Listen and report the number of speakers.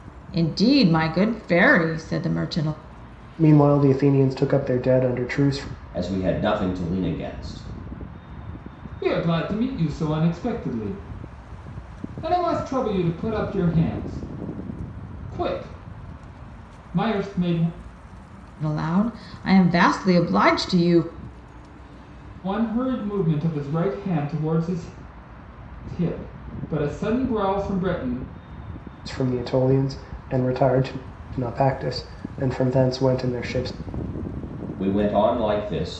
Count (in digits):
4